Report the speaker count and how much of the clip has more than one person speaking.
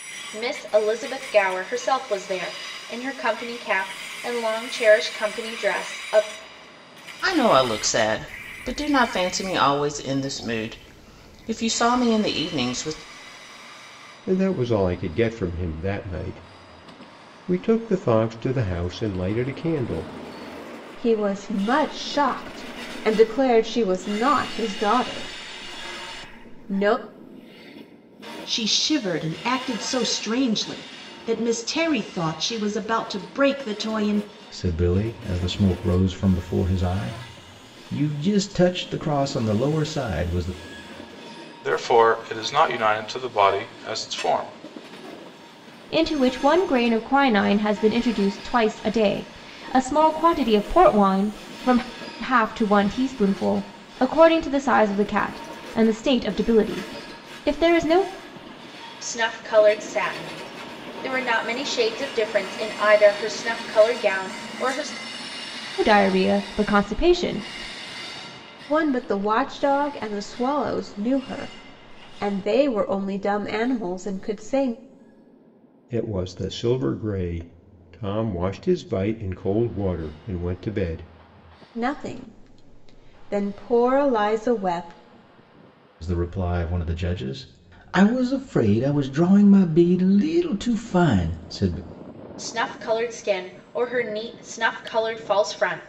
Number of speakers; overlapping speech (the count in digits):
8, no overlap